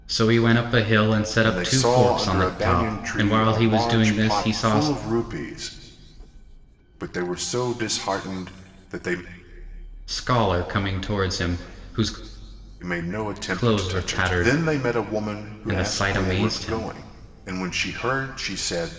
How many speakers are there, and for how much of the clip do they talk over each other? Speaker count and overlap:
two, about 31%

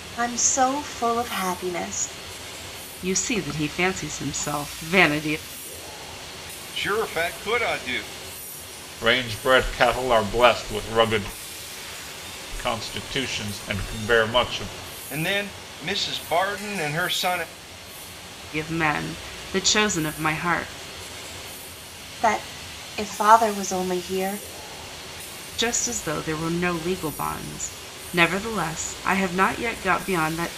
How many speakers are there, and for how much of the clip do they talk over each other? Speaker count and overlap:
four, no overlap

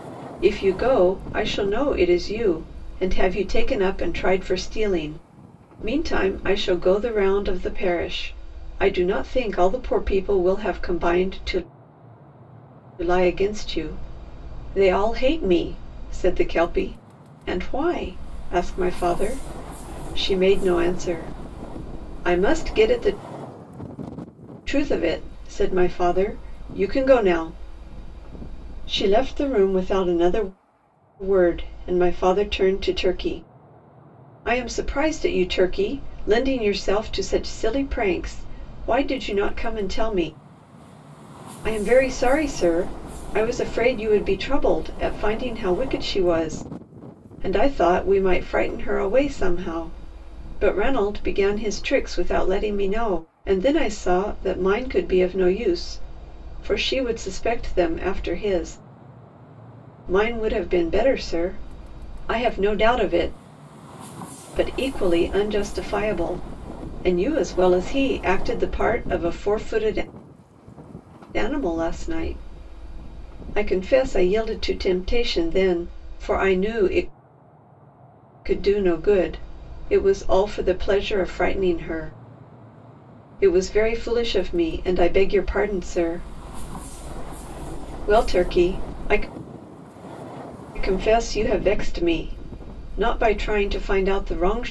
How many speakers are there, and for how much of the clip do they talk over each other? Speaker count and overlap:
one, no overlap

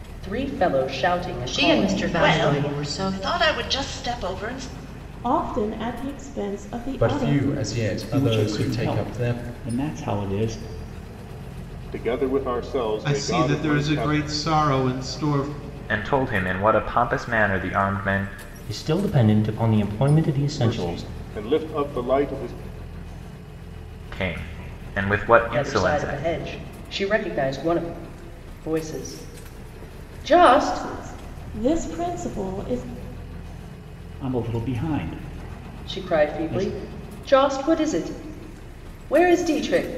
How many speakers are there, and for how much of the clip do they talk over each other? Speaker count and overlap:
ten, about 18%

